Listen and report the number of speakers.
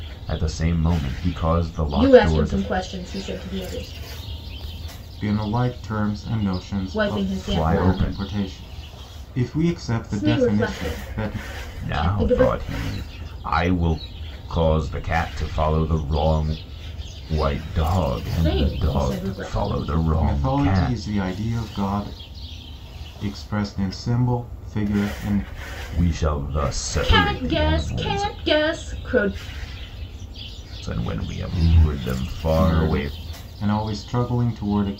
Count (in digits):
3